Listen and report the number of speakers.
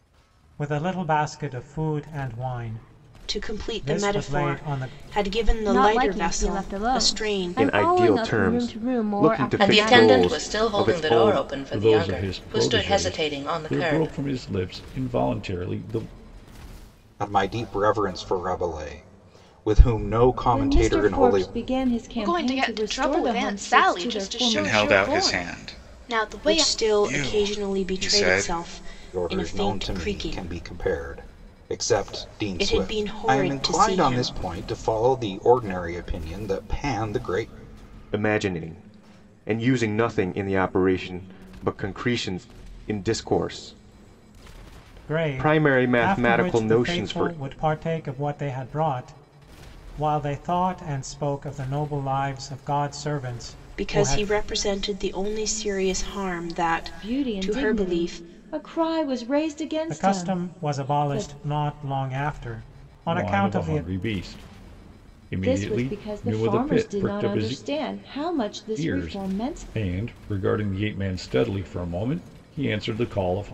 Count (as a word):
ten